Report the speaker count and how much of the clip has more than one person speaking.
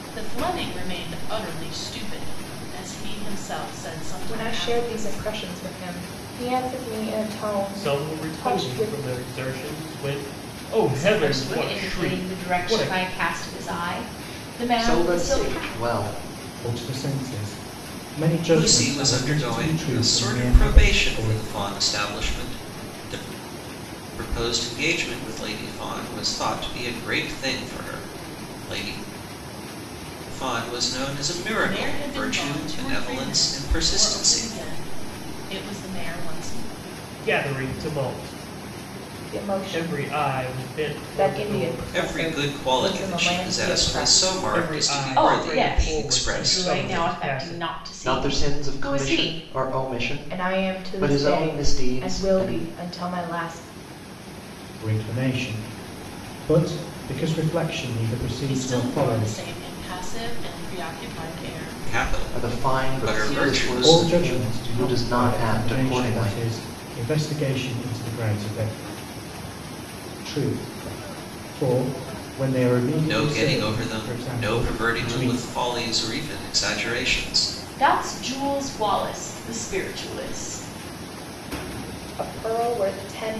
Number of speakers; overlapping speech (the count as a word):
seven, about 38%